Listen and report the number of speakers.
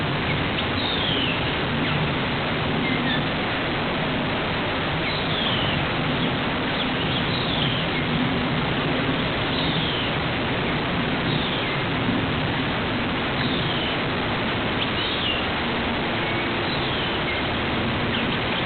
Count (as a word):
zero